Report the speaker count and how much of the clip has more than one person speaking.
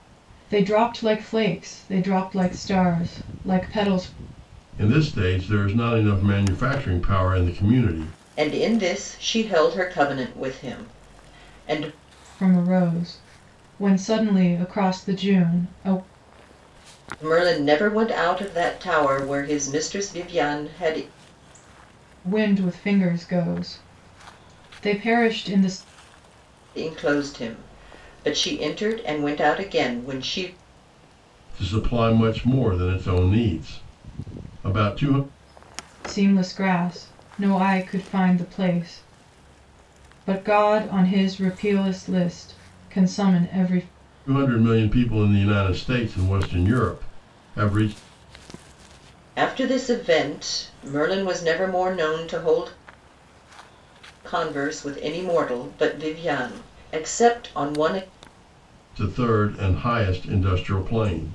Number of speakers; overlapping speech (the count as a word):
three, no overlap